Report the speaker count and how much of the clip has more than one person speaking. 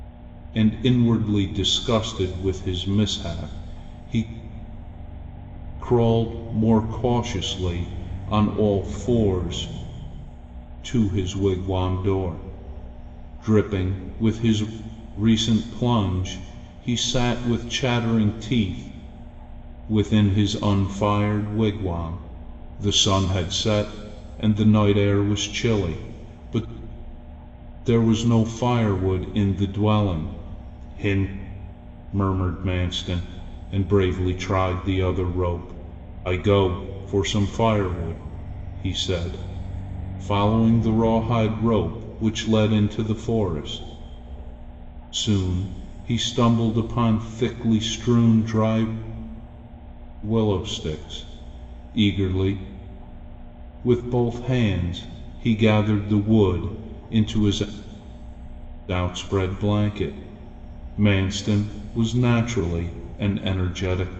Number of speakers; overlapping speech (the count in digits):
1, no overlap